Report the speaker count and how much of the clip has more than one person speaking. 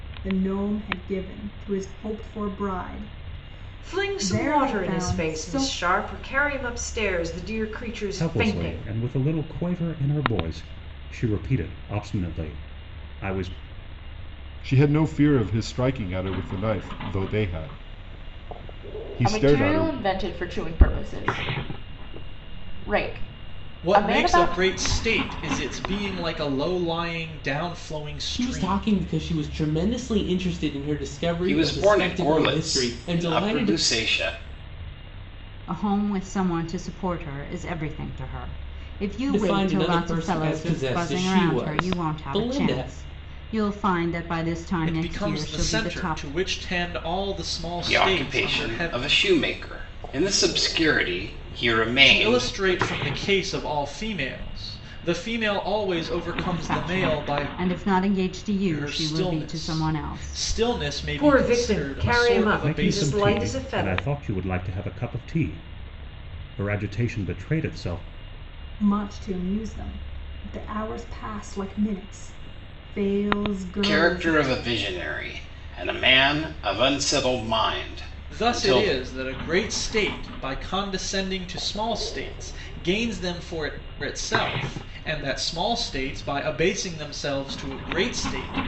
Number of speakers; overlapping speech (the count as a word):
nine, about 25%